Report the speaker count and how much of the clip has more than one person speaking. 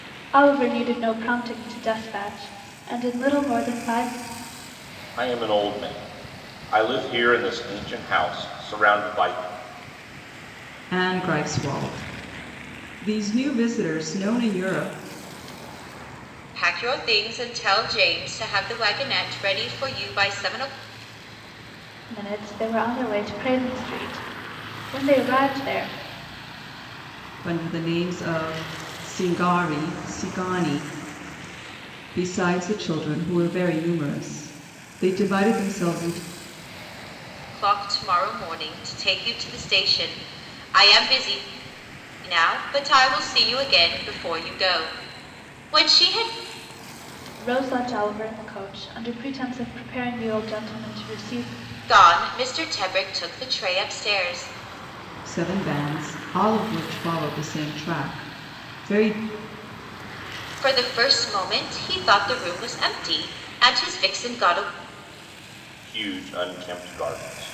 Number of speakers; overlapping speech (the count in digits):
4, no overlap